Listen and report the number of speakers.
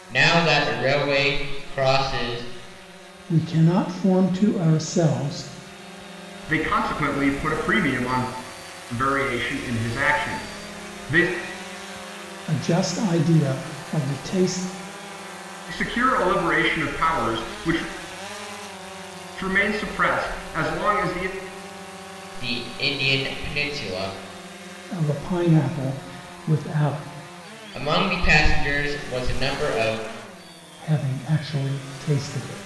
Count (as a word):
three